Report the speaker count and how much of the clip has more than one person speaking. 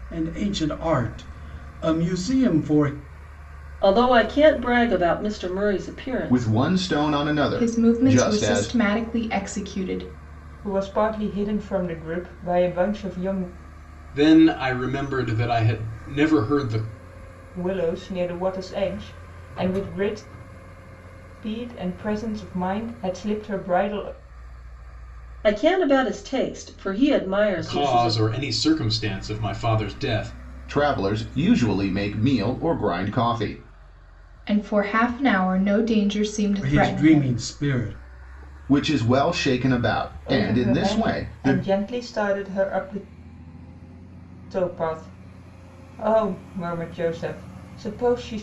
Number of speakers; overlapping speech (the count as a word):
six, about 9%